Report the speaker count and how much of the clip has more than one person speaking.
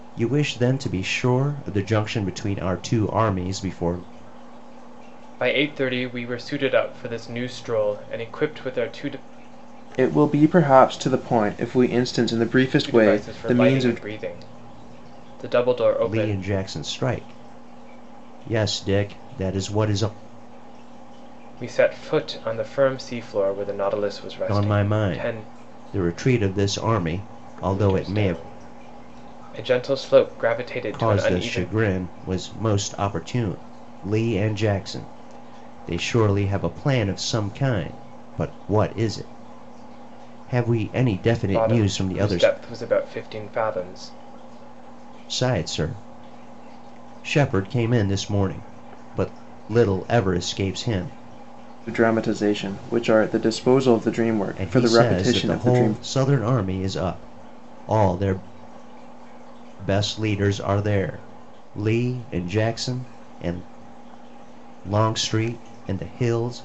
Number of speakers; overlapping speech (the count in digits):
3, about 10%